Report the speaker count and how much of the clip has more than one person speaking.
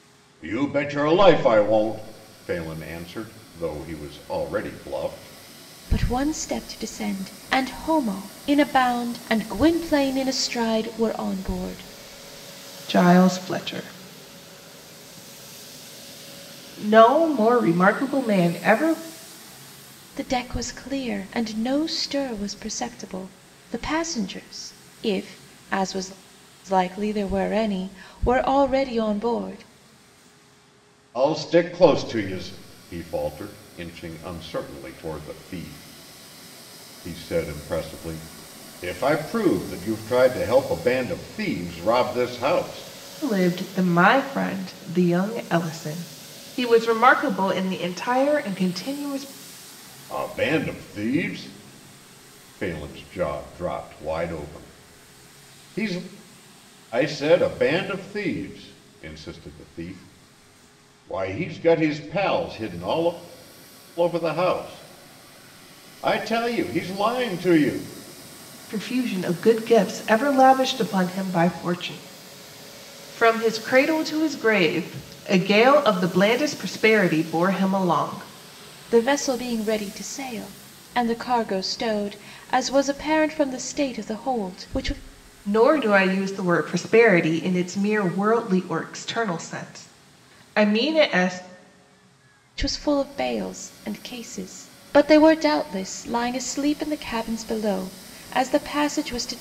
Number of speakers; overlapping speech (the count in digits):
3, no overlap